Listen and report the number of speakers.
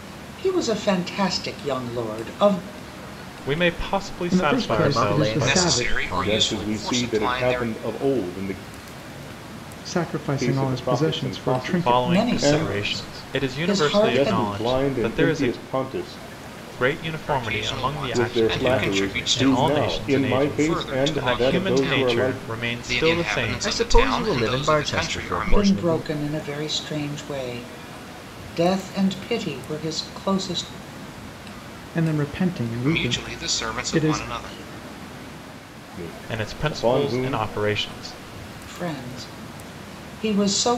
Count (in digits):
6